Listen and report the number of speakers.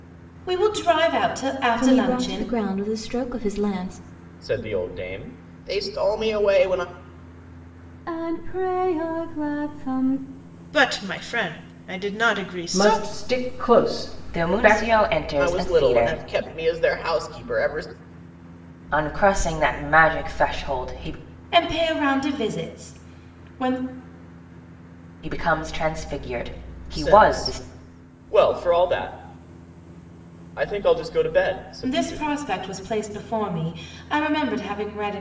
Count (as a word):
seven